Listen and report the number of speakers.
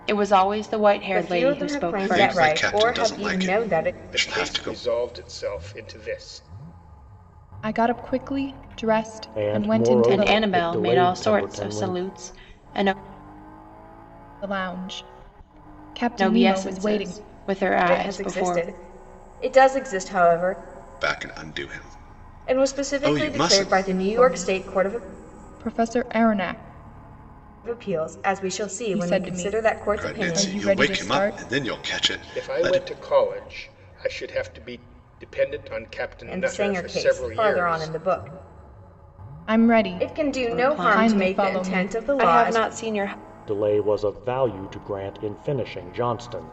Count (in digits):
6